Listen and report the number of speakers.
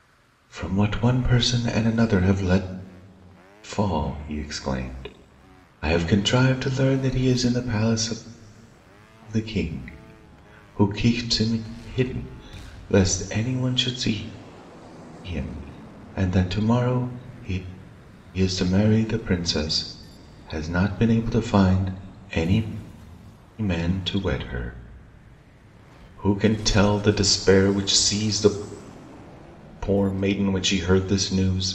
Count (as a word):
one